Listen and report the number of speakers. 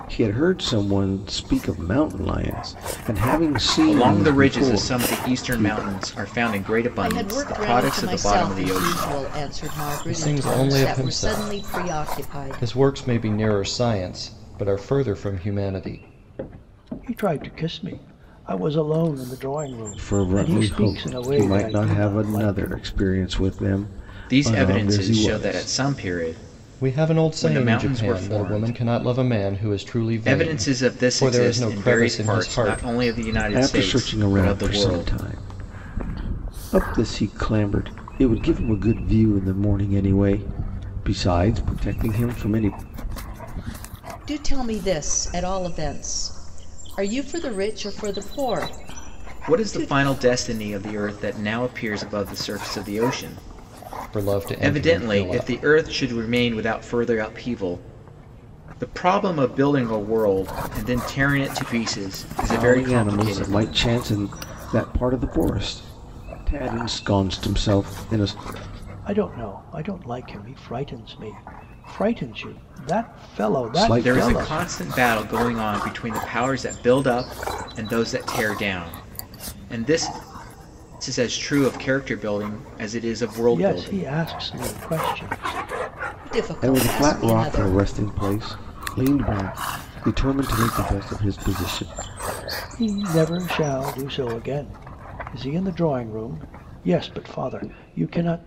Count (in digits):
5